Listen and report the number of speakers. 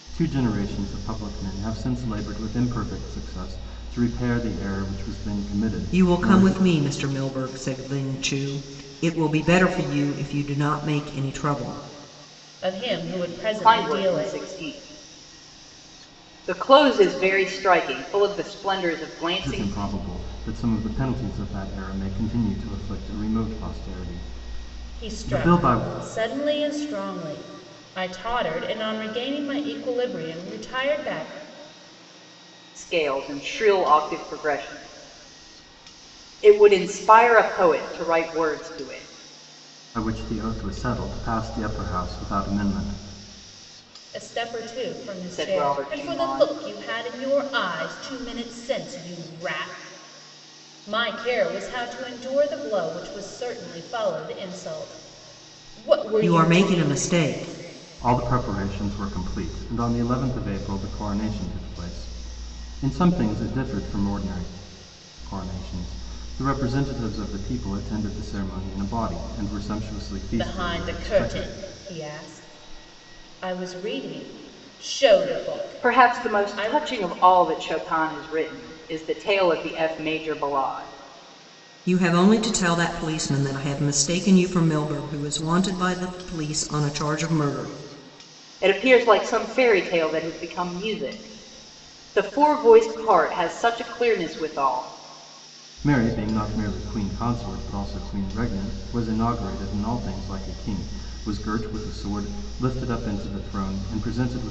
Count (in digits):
4